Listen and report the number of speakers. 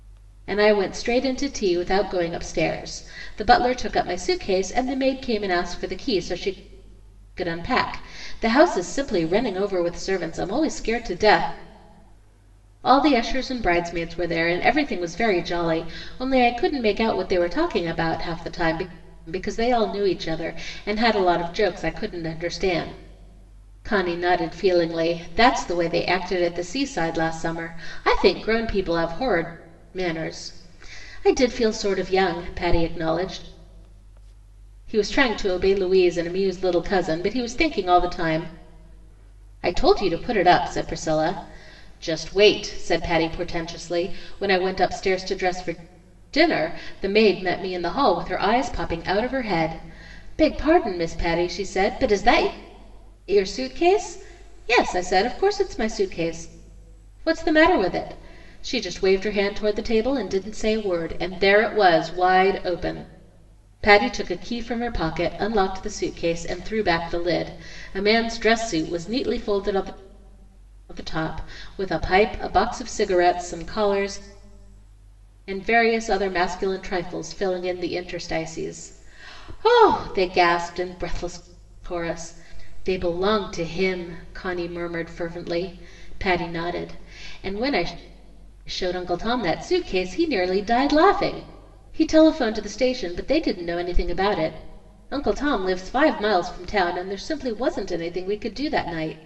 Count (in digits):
1